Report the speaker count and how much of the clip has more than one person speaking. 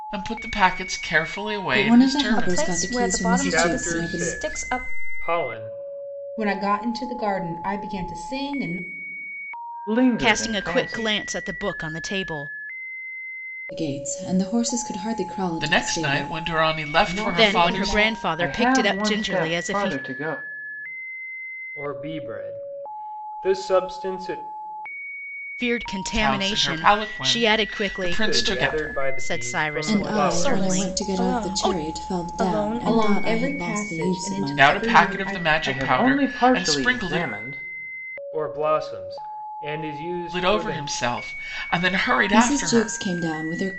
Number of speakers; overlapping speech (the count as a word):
seven, about 45%